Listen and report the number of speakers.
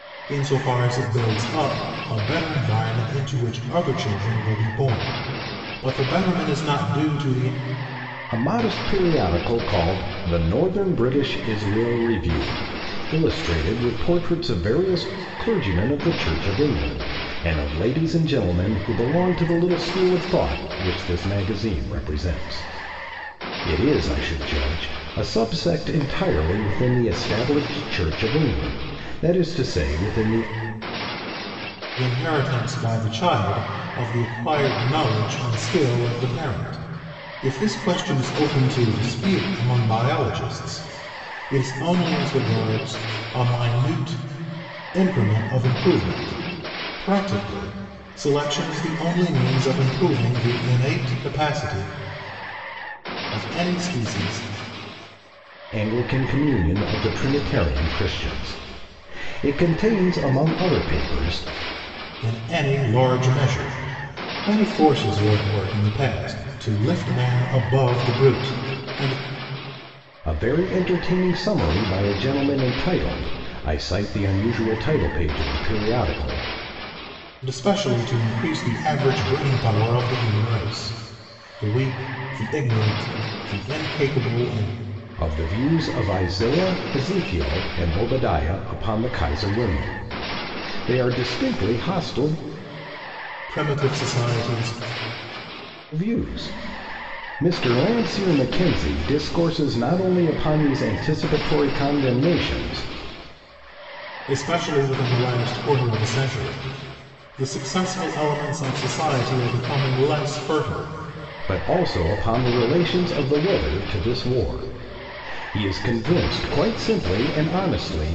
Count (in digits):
2